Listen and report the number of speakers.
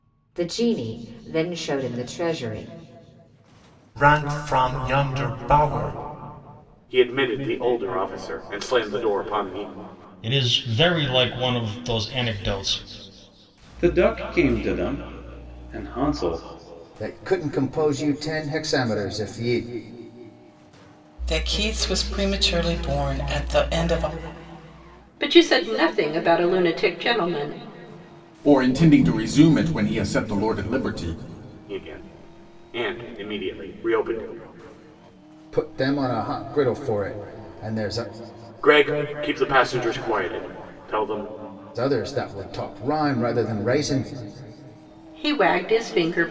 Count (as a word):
nine